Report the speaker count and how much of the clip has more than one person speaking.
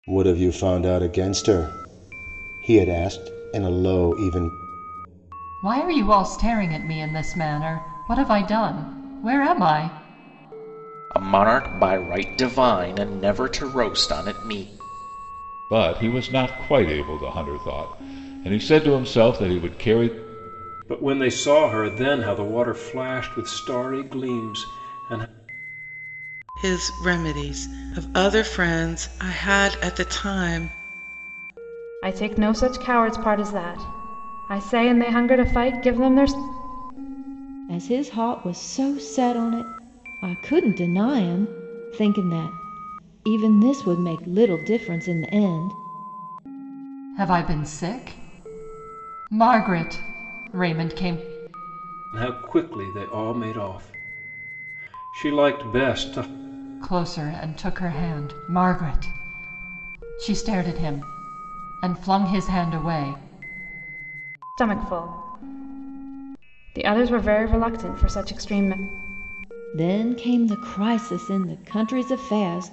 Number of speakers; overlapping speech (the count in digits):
8, no overlap